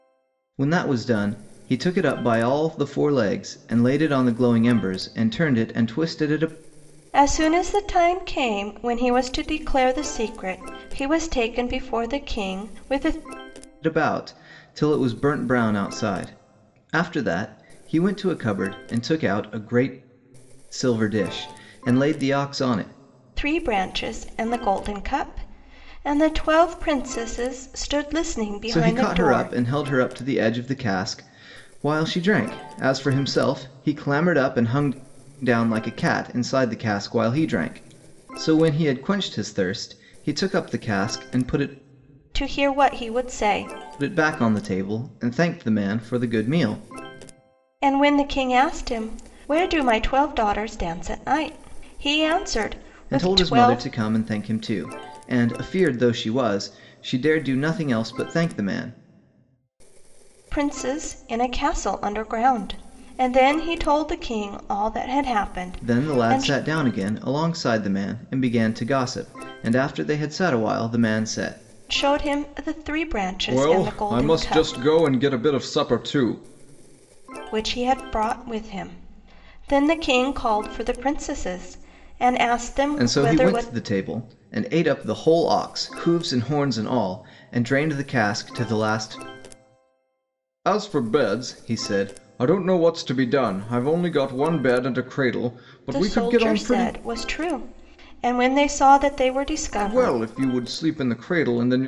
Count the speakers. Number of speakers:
2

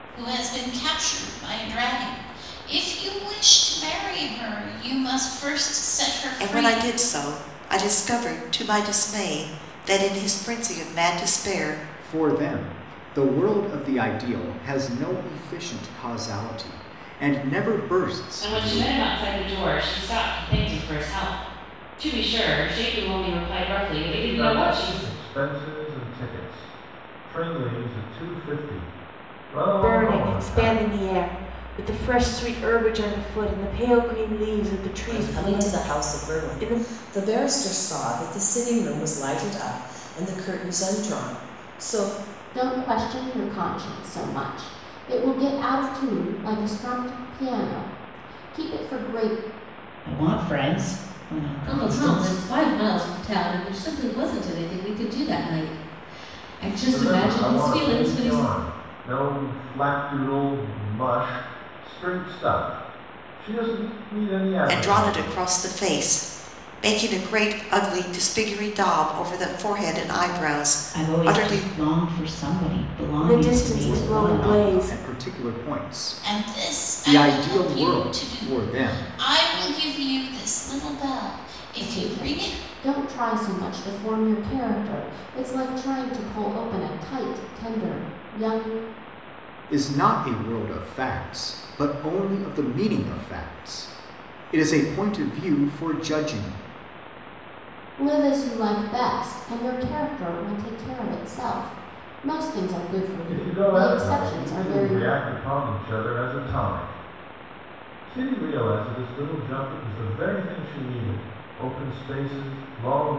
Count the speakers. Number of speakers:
10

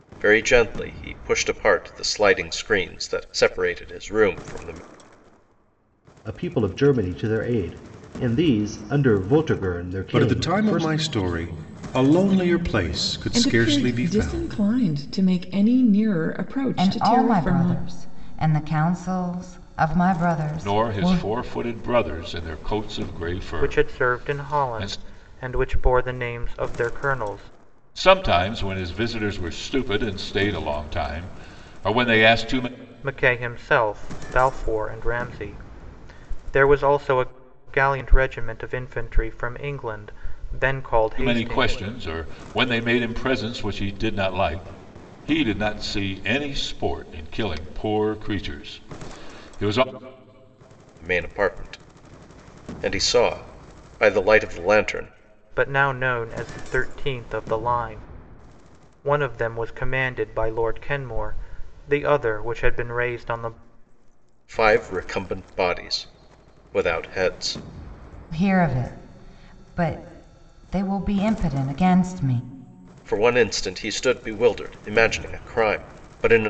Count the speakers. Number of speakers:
7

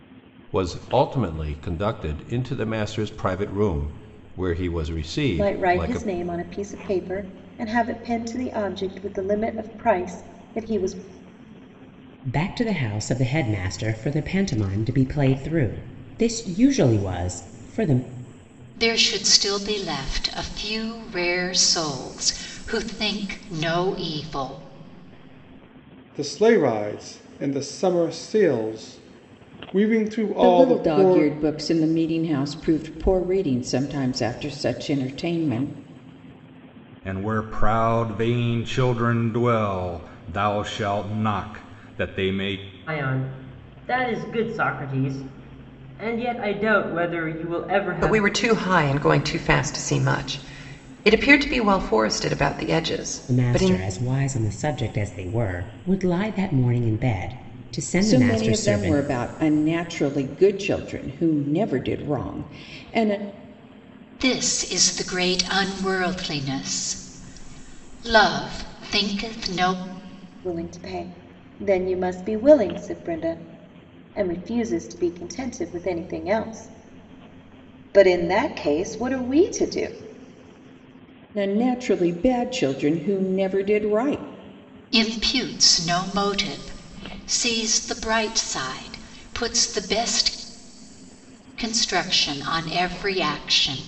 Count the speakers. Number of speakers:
9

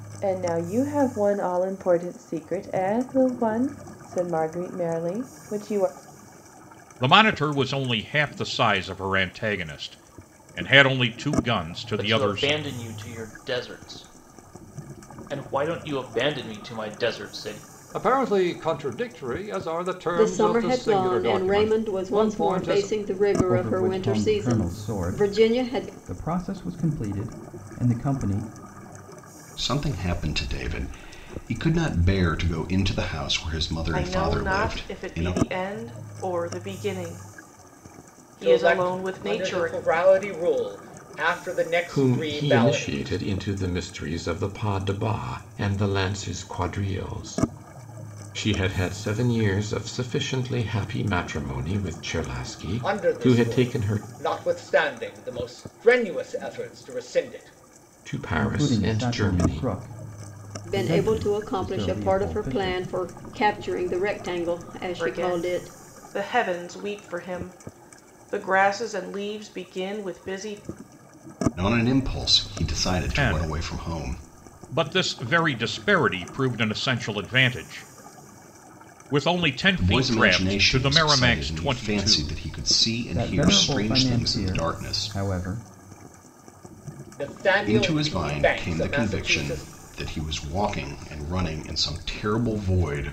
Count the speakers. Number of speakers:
10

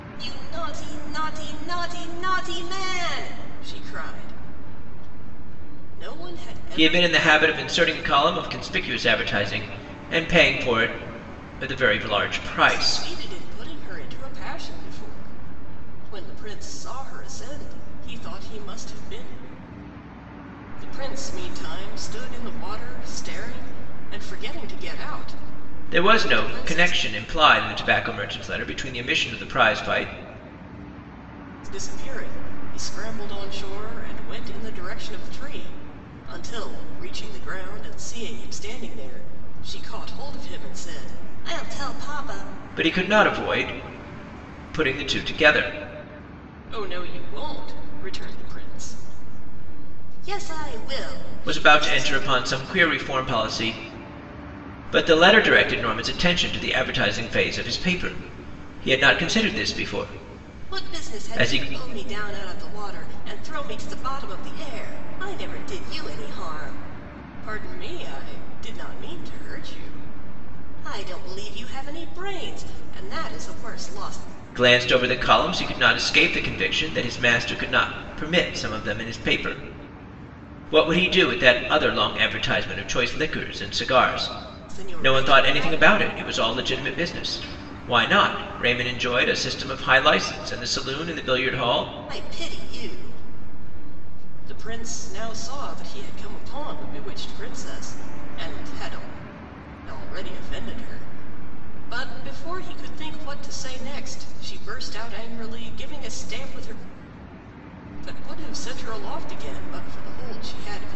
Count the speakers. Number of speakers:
2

